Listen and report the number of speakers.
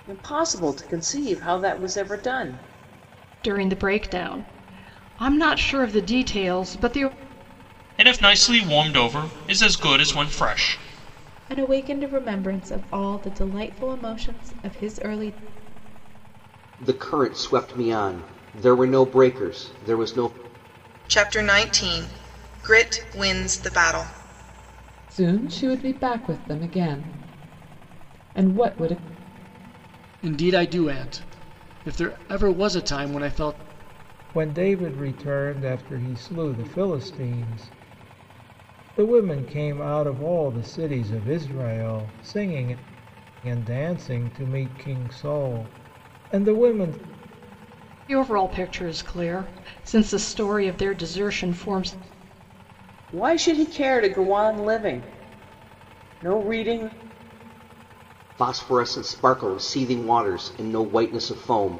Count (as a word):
nine